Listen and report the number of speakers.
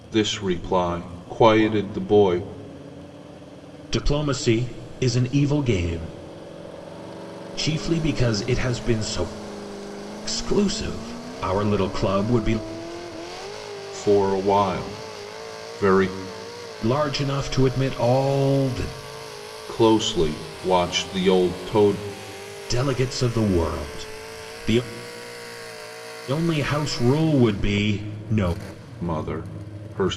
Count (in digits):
2